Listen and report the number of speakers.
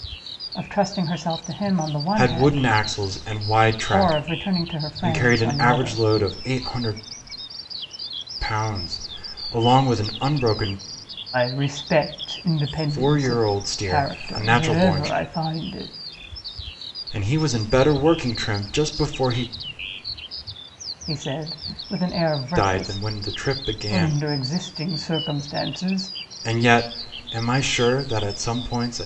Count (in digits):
2